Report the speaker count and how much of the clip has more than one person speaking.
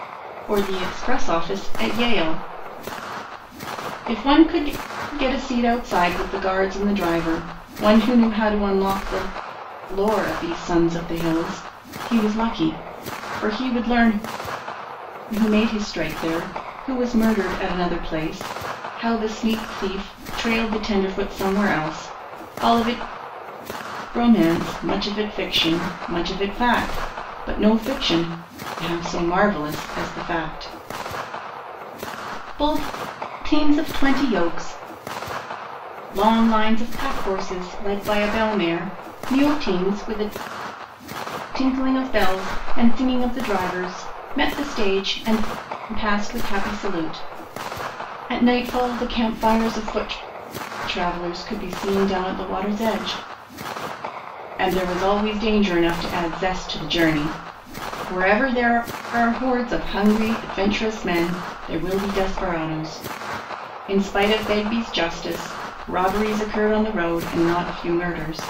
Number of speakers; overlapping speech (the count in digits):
1, no overlap